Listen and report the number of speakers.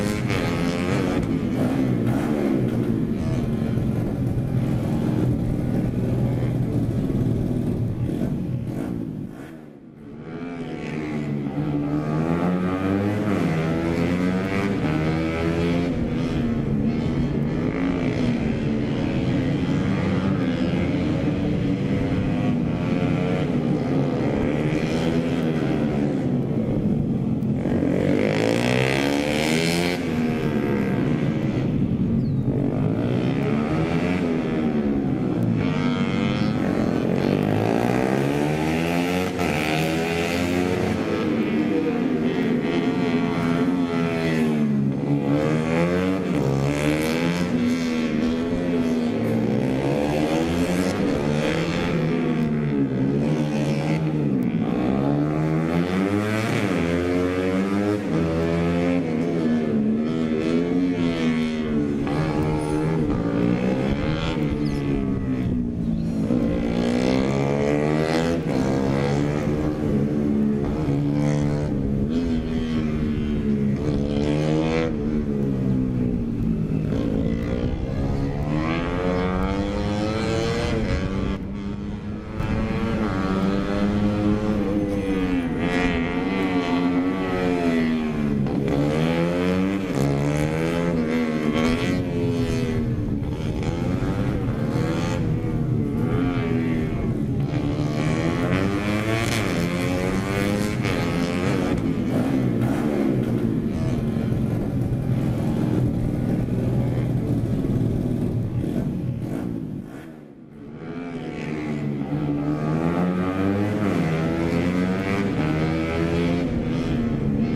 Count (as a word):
zero